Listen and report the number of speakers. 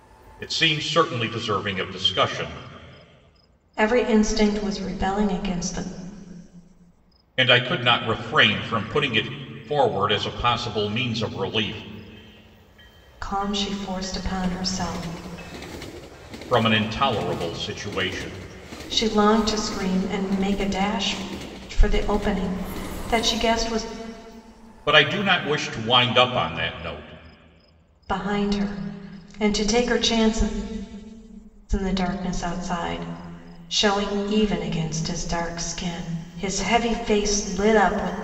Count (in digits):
2